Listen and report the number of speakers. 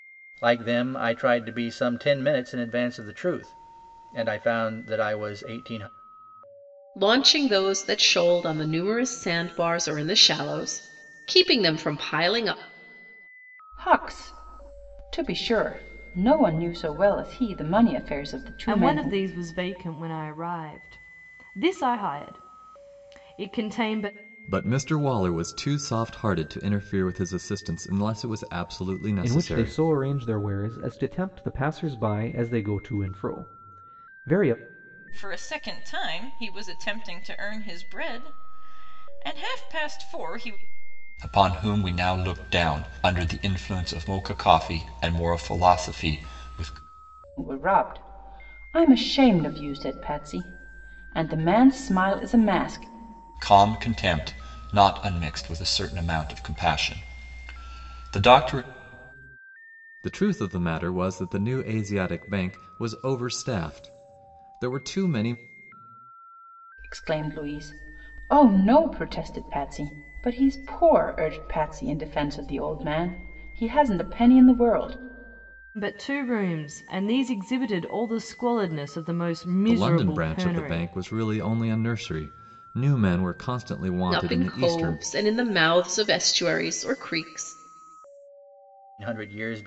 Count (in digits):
8